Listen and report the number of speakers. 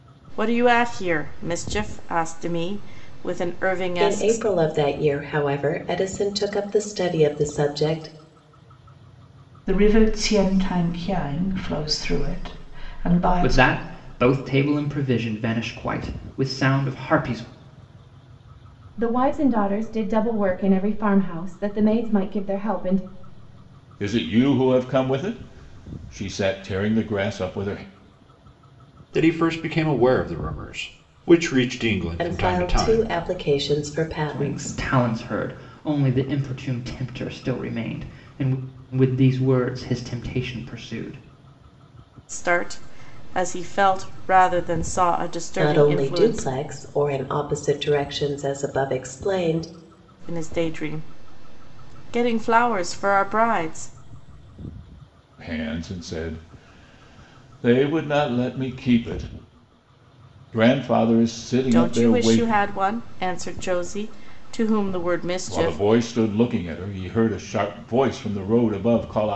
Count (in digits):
7